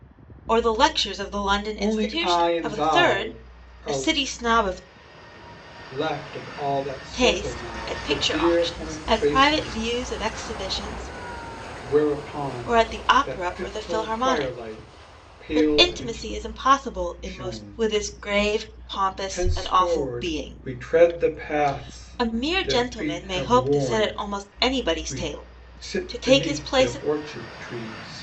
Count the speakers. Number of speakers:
two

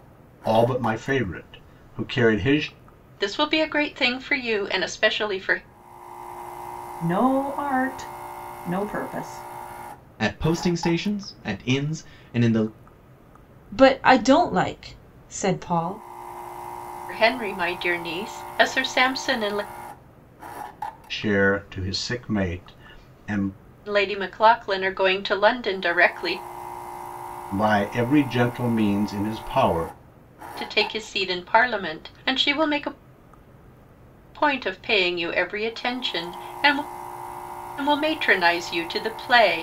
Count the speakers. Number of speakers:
five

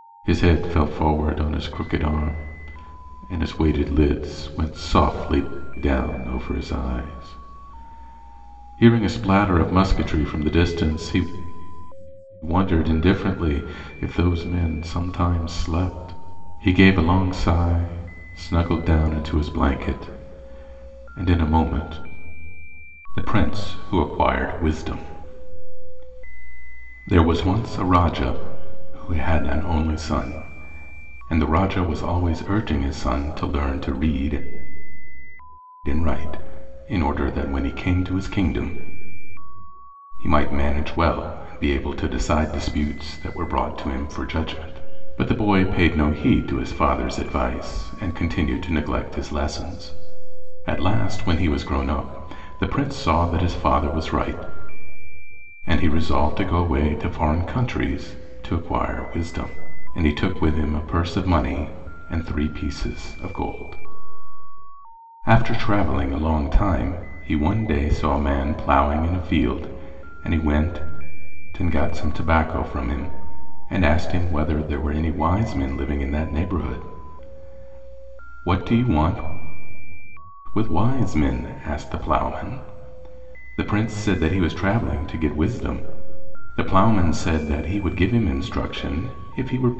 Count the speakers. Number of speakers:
one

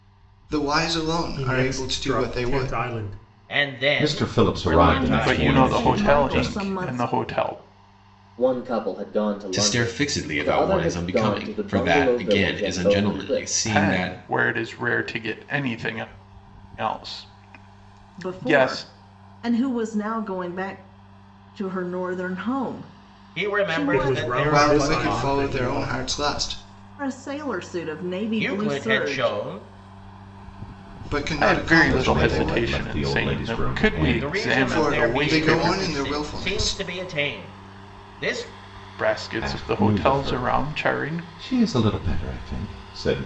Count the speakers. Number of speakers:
eight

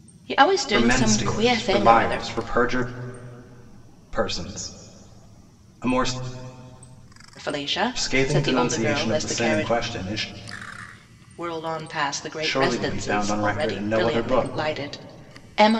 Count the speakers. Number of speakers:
two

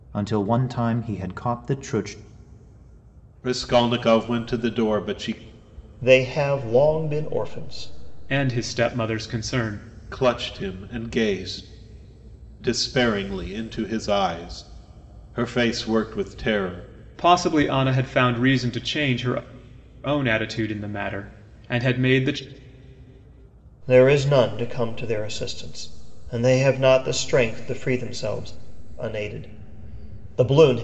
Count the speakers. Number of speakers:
four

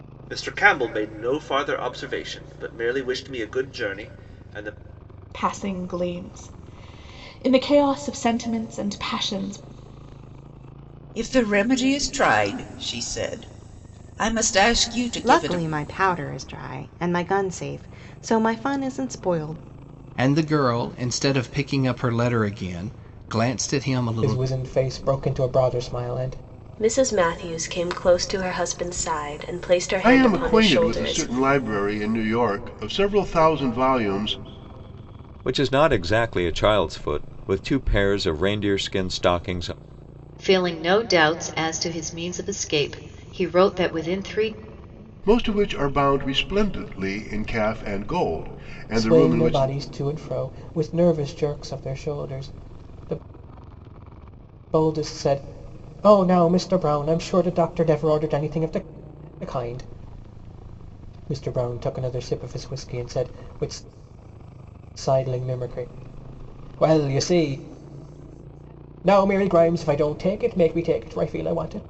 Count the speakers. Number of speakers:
ten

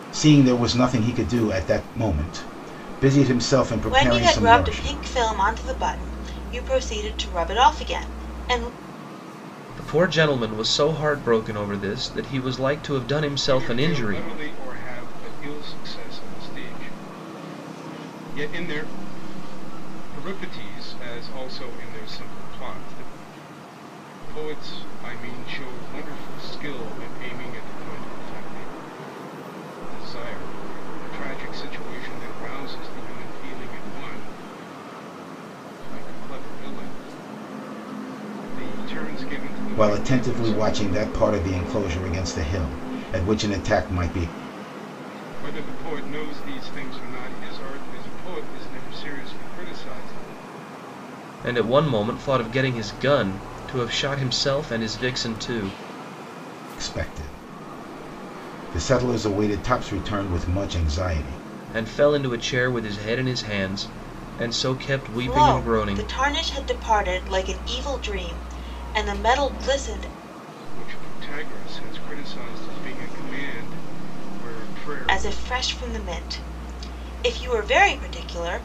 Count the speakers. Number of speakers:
four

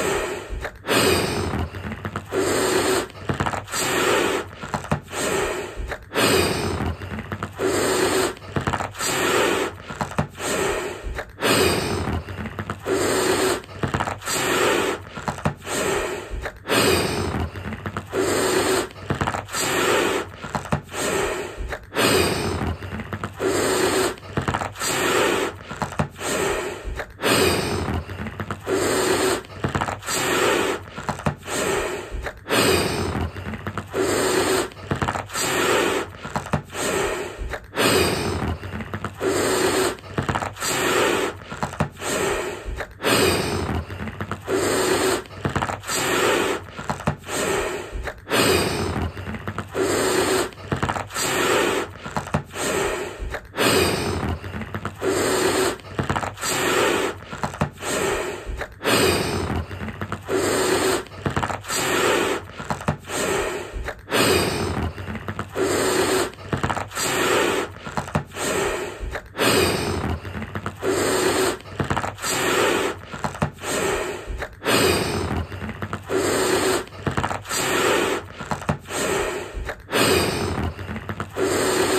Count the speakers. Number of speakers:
zero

